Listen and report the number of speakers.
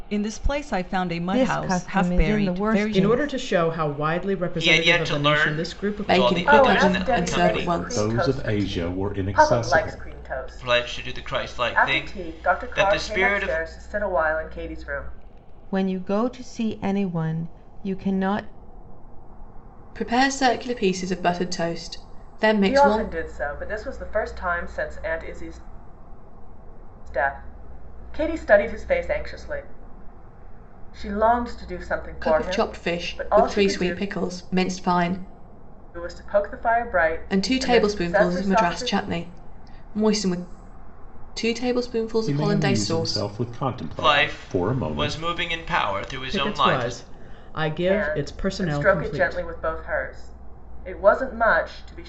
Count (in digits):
7